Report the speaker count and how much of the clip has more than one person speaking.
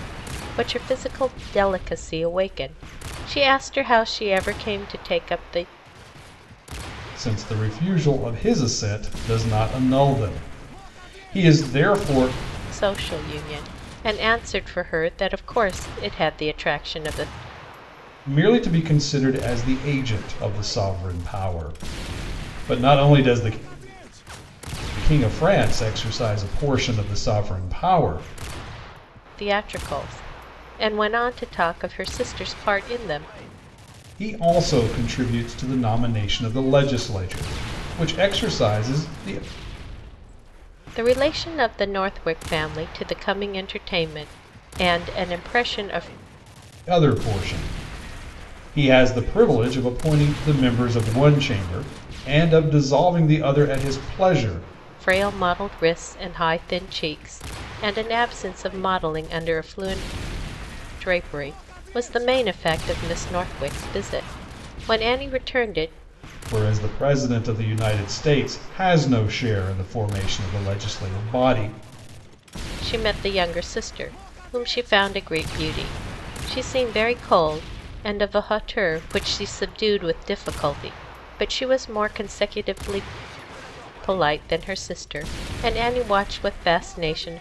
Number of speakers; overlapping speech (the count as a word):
two, no overlap